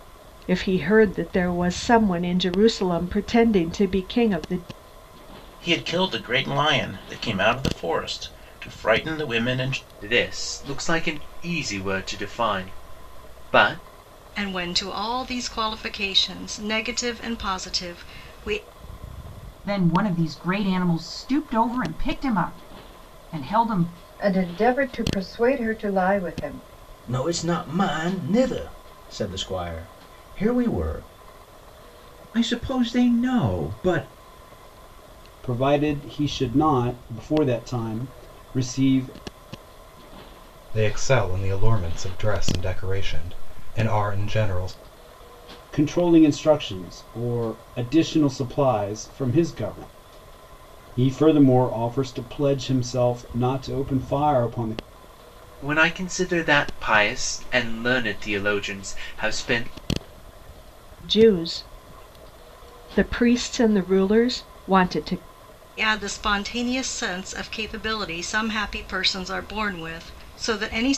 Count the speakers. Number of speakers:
10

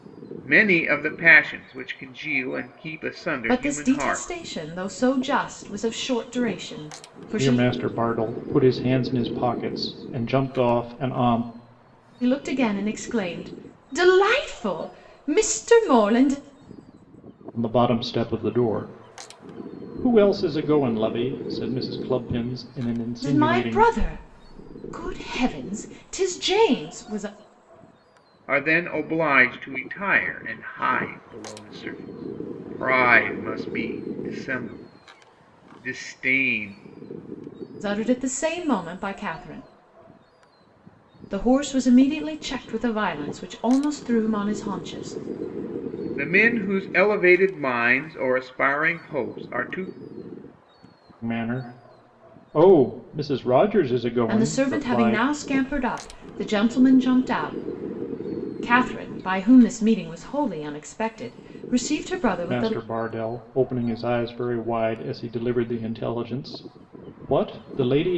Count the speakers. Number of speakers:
3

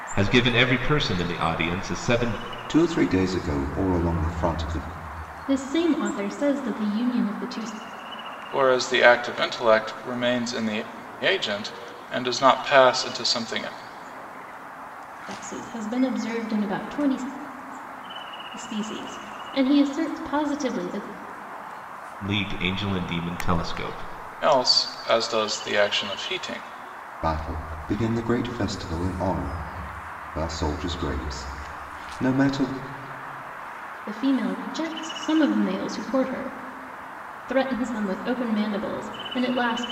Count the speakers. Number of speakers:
4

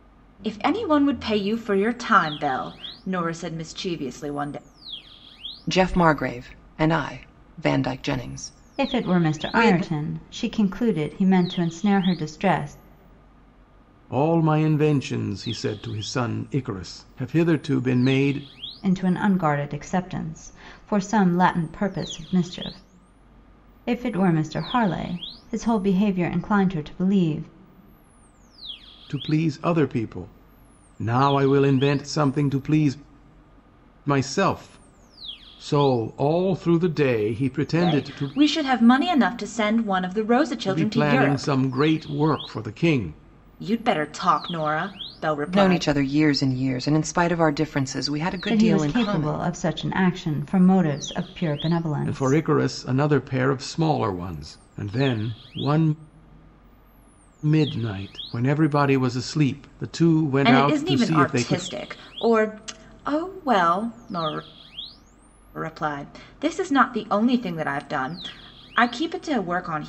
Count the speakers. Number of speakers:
4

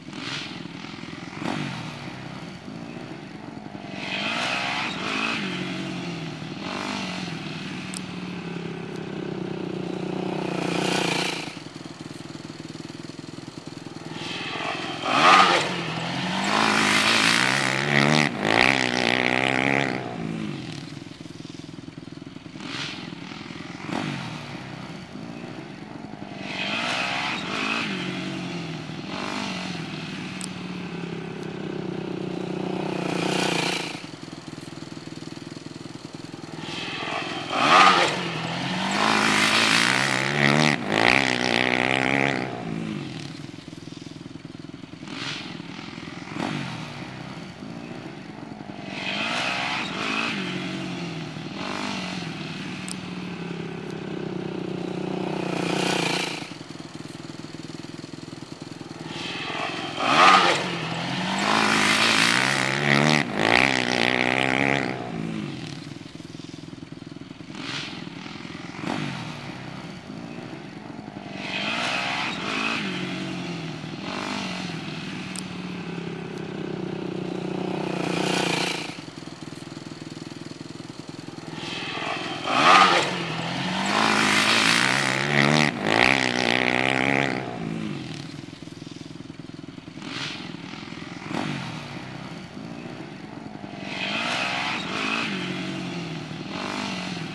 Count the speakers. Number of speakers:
0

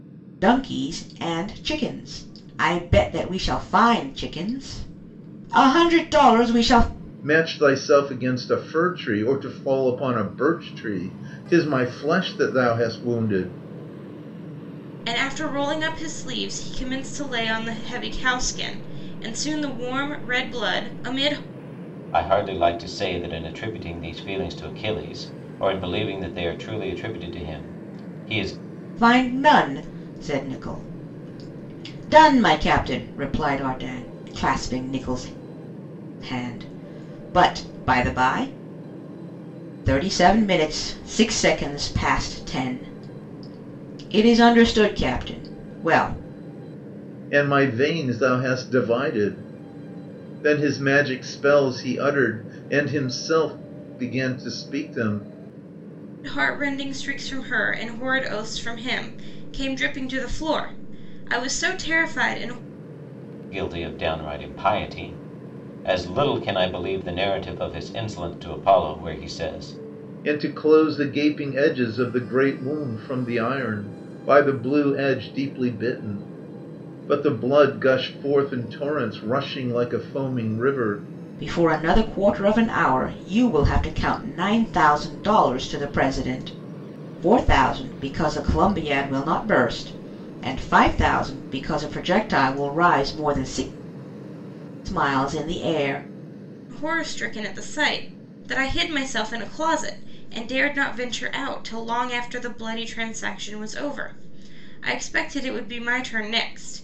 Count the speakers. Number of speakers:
4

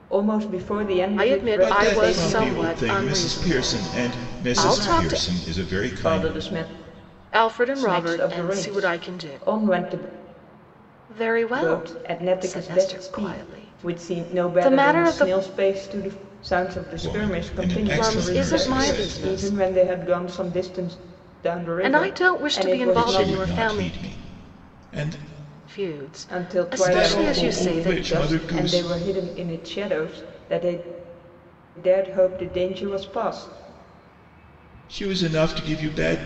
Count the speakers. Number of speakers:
3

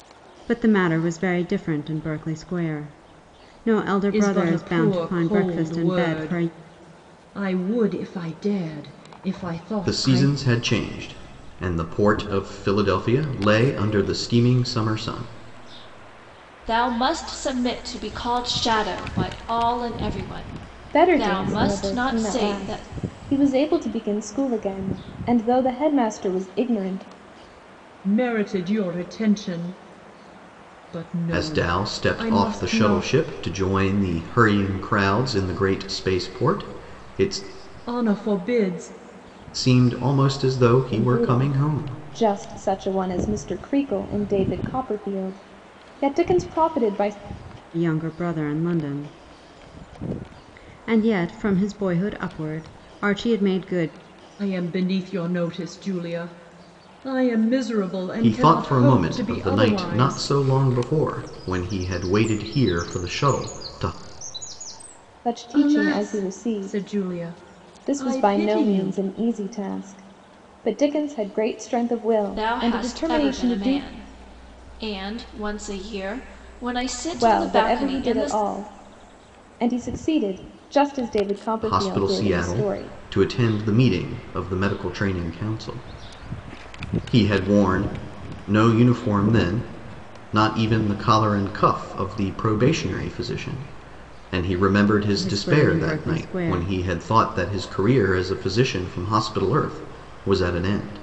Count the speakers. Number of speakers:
5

